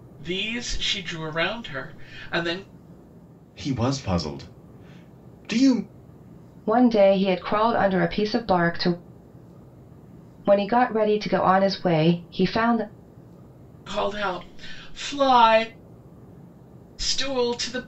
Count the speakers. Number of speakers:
three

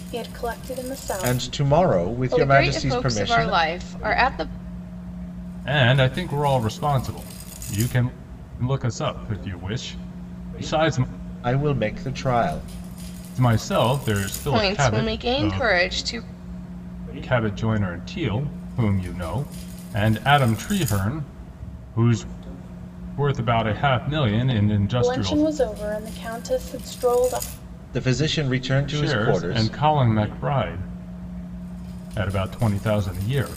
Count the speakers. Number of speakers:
four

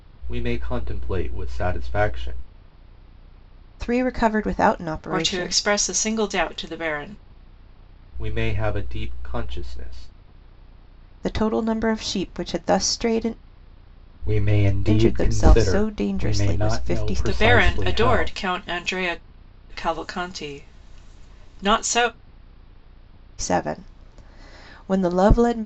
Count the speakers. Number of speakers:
three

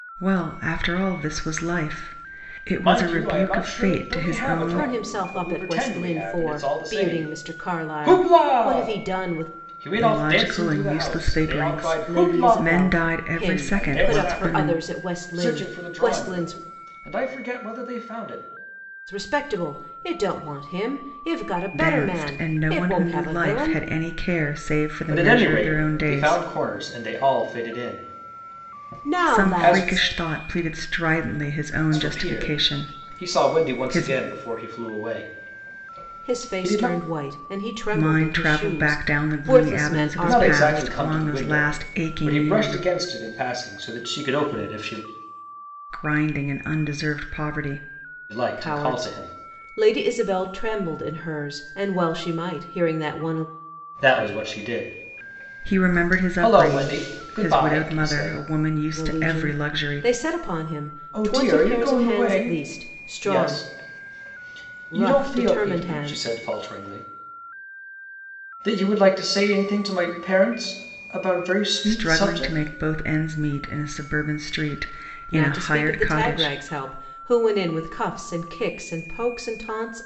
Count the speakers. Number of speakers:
three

